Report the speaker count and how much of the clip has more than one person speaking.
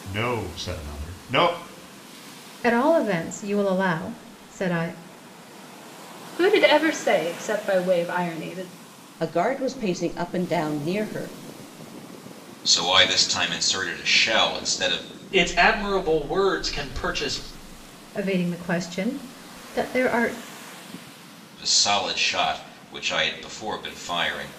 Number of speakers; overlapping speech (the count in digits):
6, no overlap